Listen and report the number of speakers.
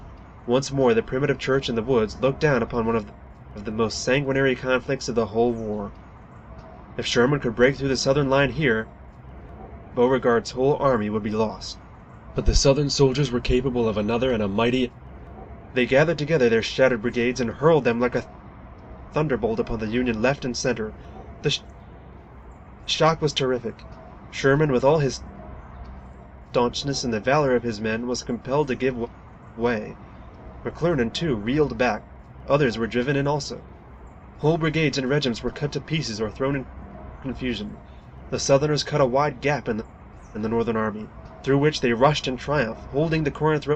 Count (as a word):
one